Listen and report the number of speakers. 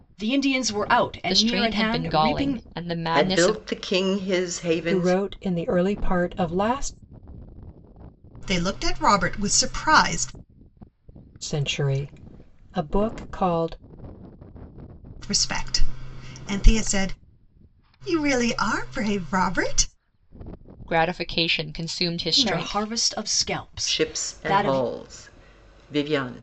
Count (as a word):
five